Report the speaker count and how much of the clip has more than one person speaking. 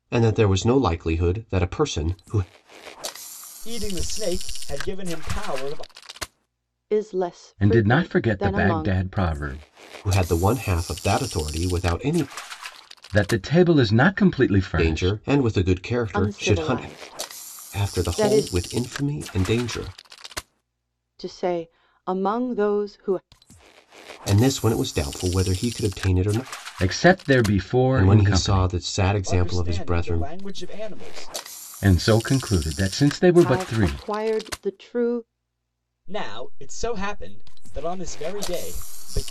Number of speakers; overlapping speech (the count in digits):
4, about 16%